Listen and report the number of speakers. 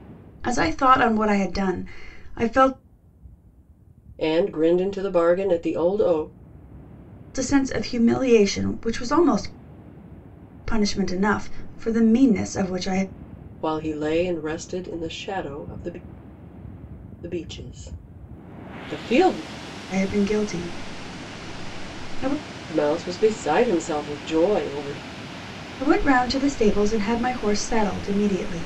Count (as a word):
two